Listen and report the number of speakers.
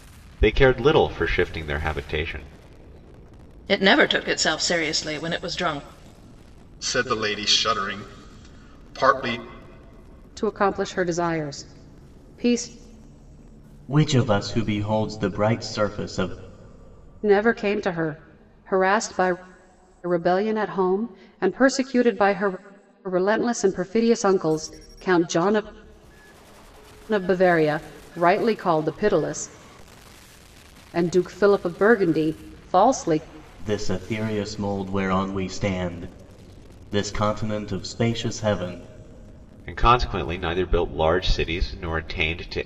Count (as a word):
five